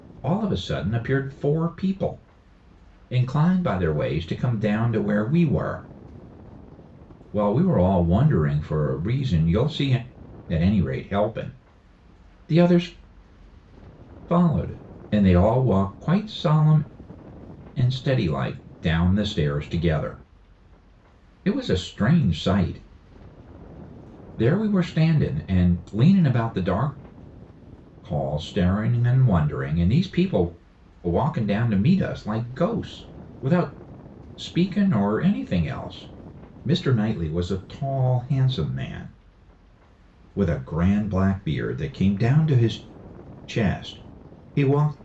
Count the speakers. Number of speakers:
1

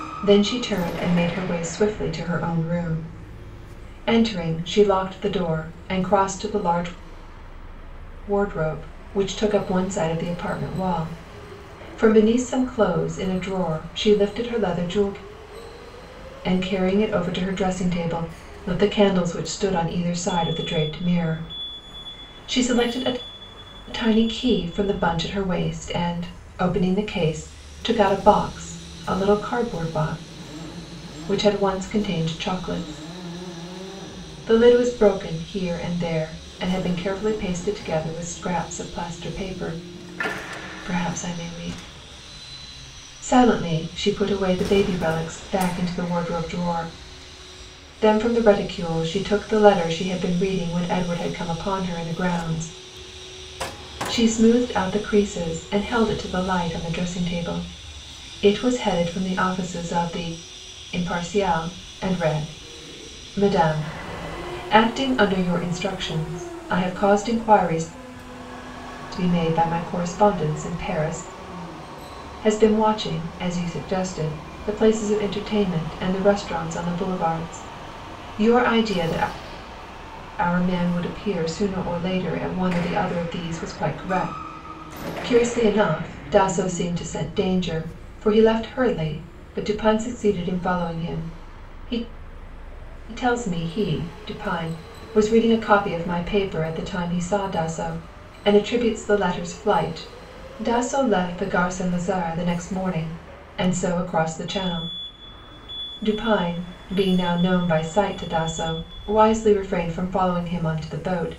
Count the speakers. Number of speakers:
1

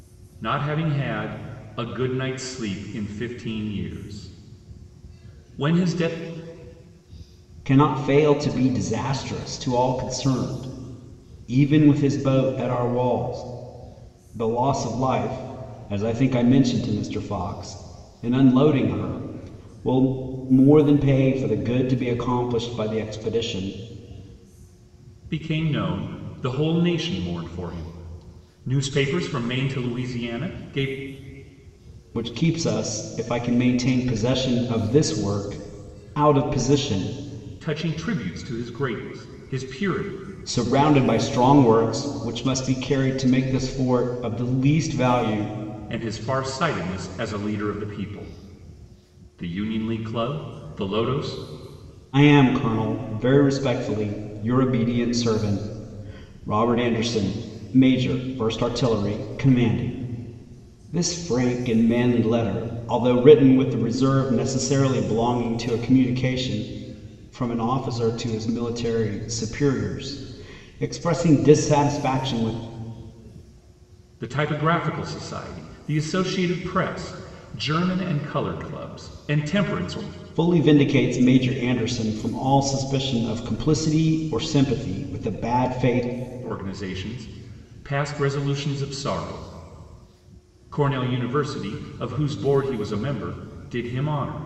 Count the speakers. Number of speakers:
2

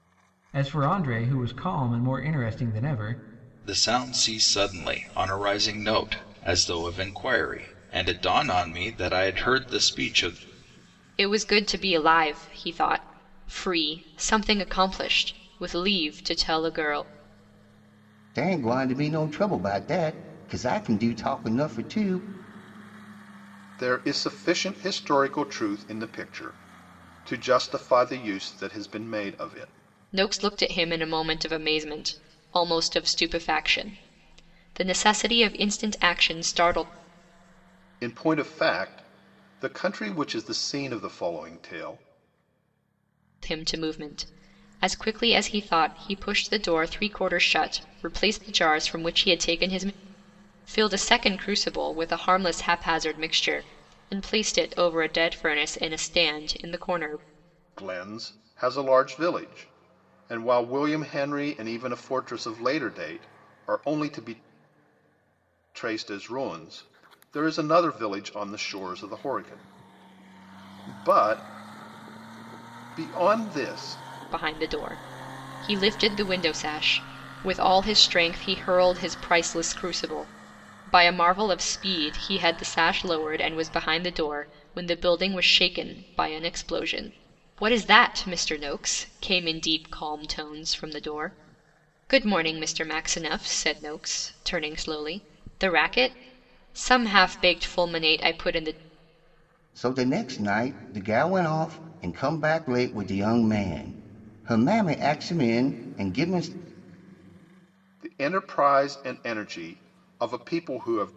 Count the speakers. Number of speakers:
5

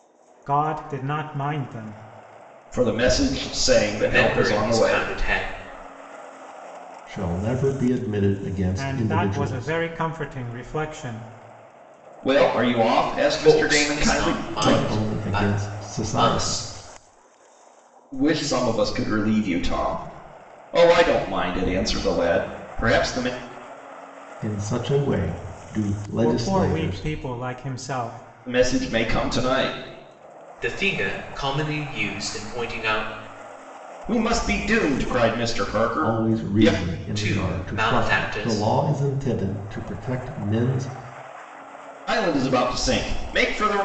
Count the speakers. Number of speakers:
4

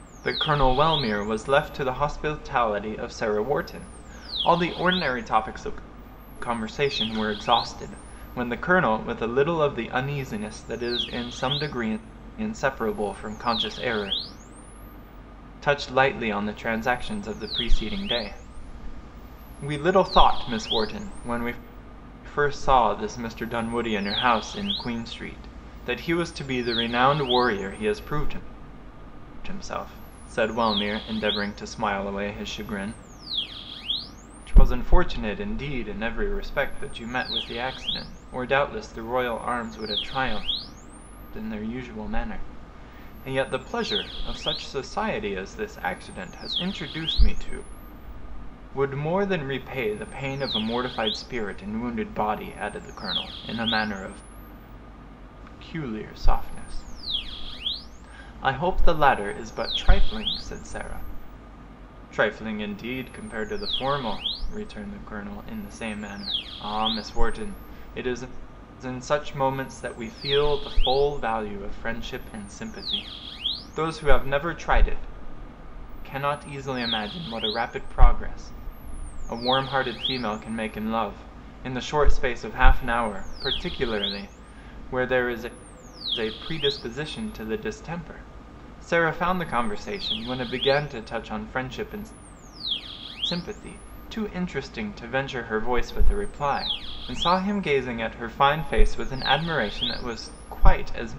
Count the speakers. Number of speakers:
1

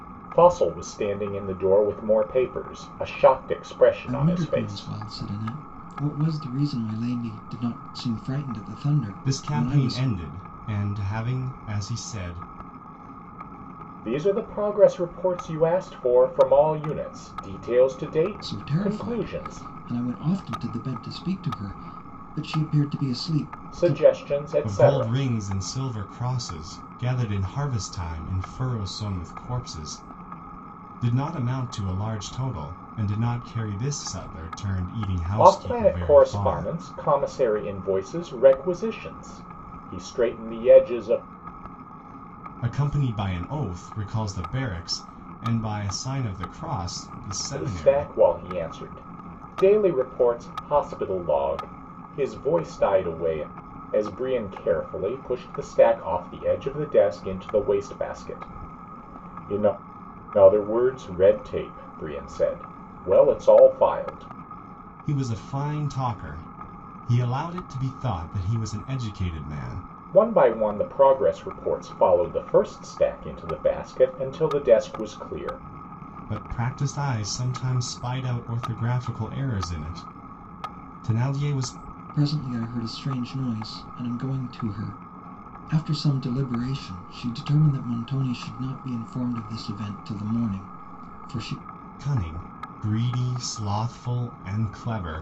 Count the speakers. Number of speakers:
3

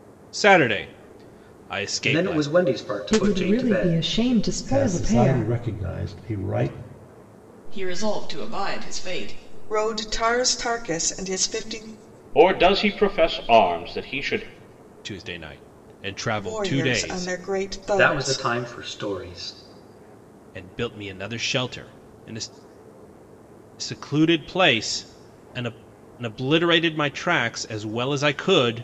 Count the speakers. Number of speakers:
7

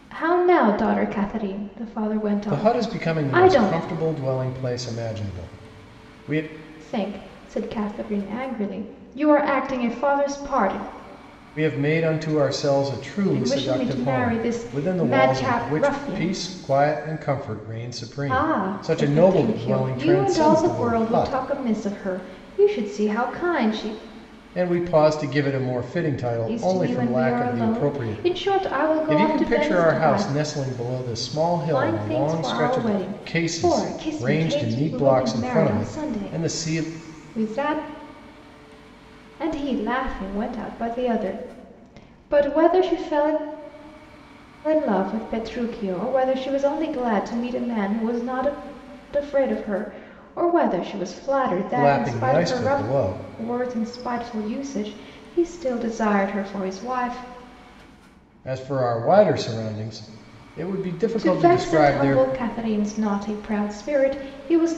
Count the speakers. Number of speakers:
2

